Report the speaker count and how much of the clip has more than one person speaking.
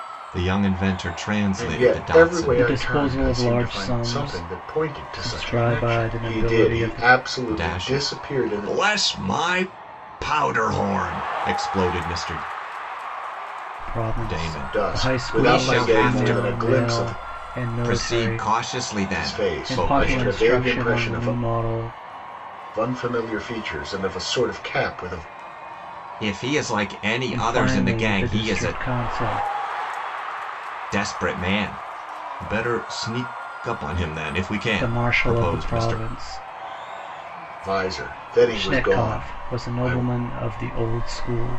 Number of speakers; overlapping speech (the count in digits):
3, about 39%